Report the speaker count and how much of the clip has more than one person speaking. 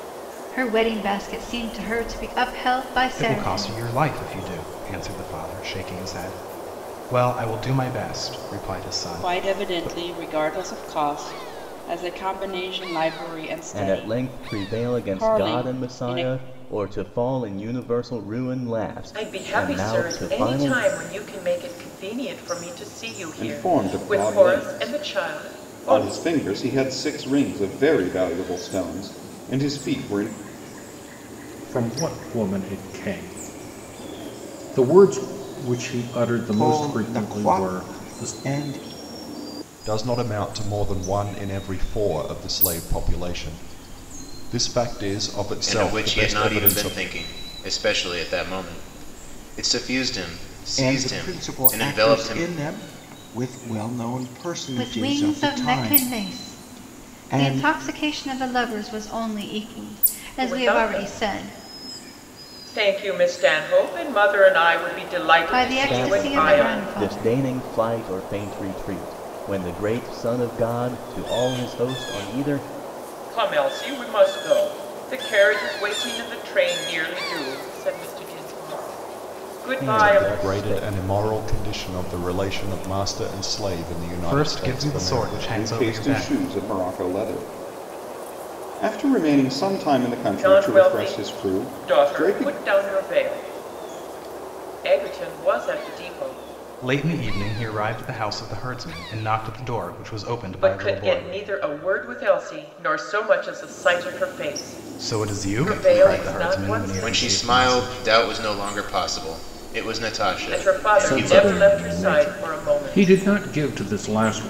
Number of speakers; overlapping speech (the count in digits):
10, about 28%